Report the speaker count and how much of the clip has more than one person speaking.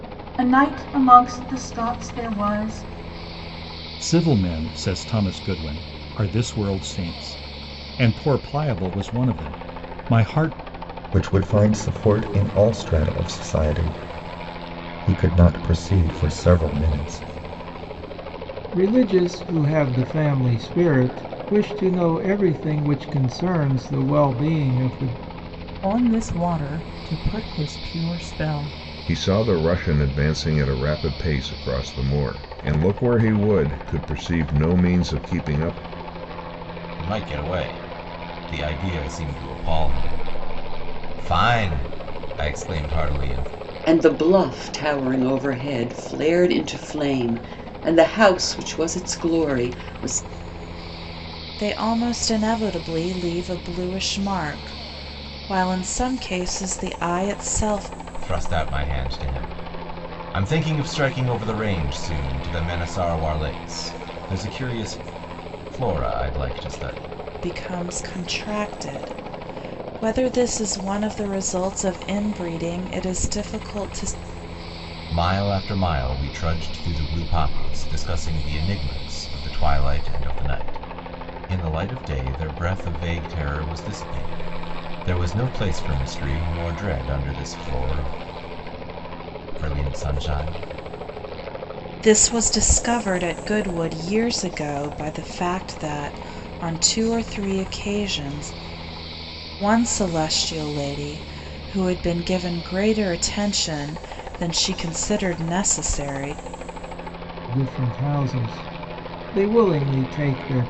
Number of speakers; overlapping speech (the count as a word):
nine, no overlap